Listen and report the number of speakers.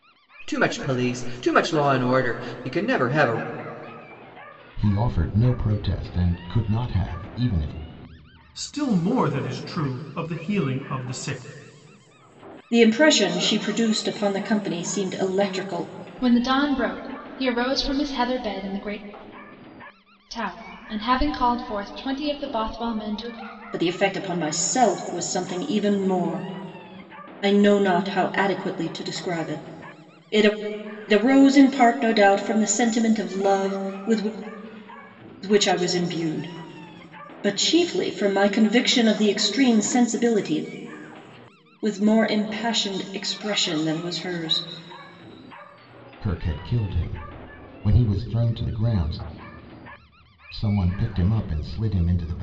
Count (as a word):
five